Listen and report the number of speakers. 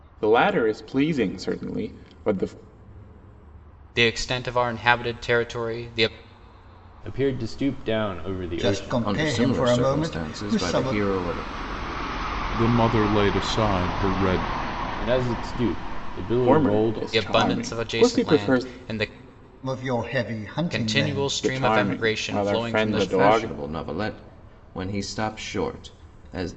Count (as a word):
six